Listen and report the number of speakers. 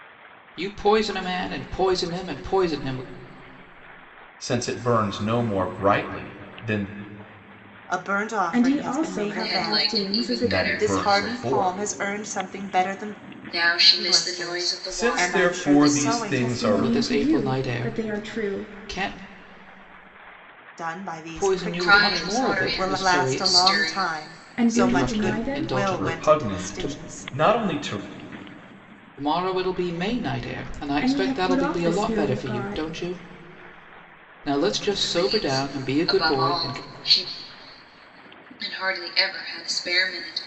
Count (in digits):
5